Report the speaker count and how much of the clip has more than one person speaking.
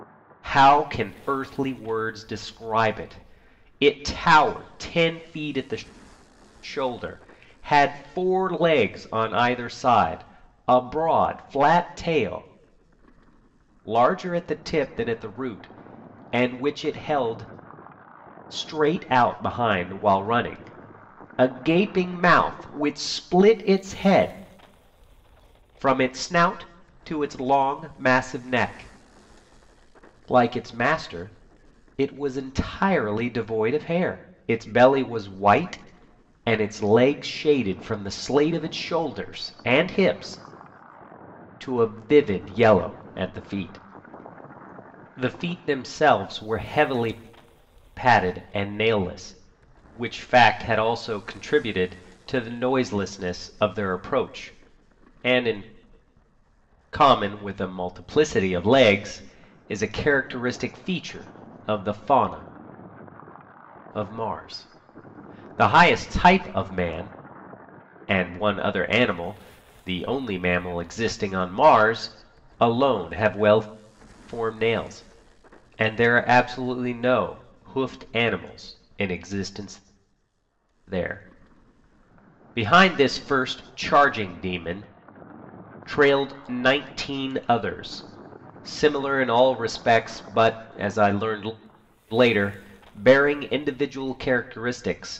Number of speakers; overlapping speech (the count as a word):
one, no overlap